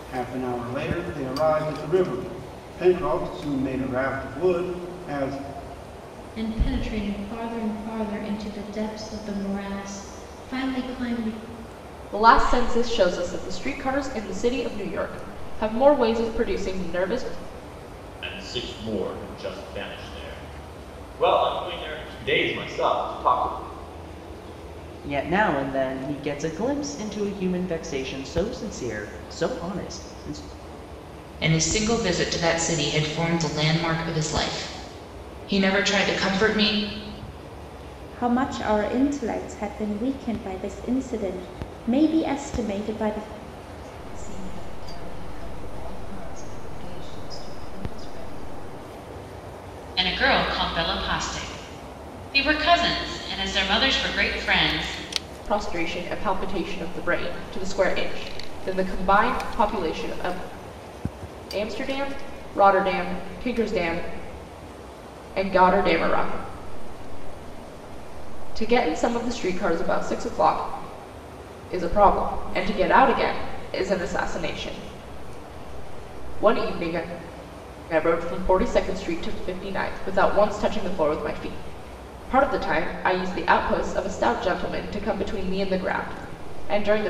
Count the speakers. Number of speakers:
9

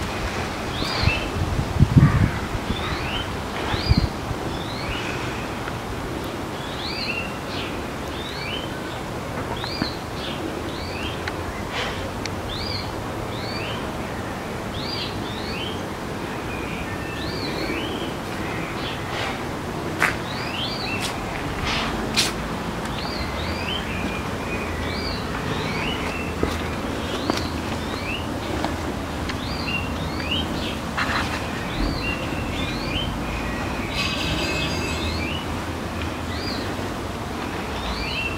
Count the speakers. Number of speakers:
0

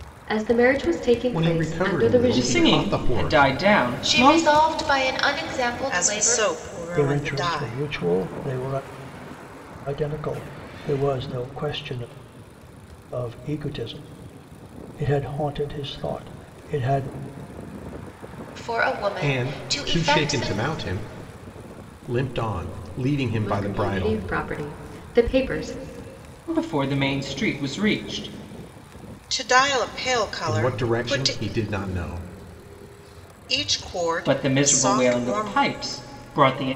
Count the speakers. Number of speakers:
6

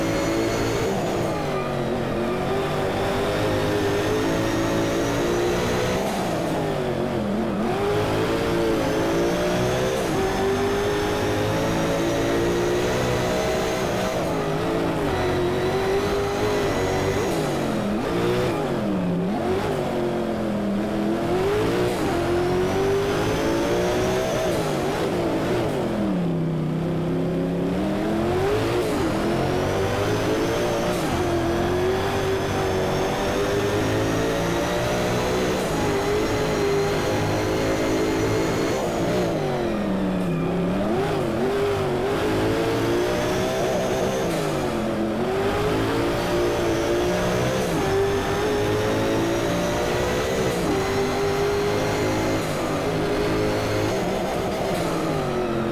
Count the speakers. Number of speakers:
0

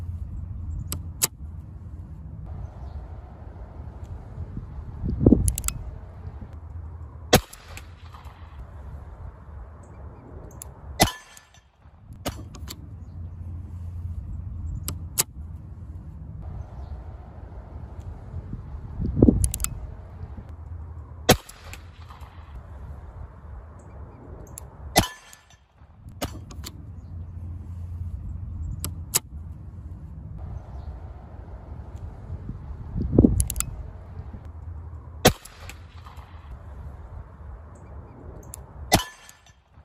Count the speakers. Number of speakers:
0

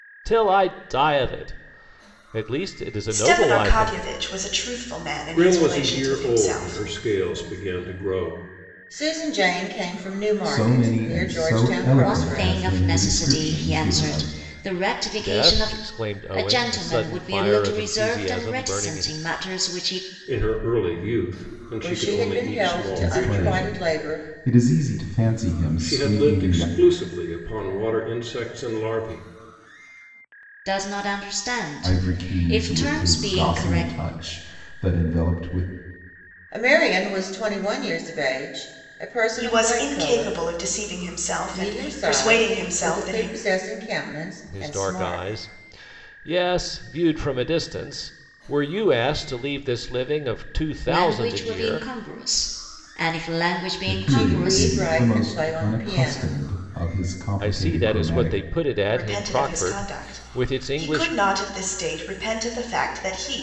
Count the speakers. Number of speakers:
6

